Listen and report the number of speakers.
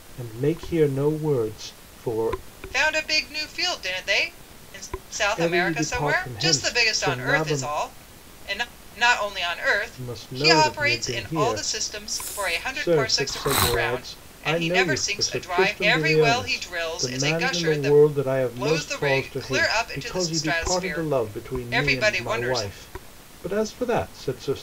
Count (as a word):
two